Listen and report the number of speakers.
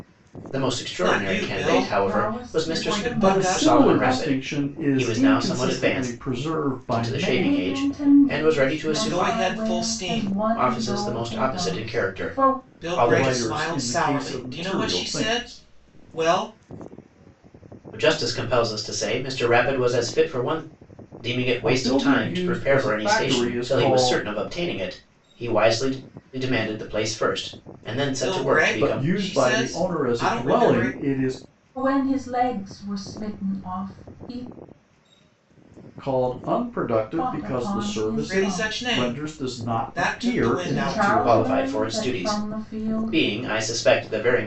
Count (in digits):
4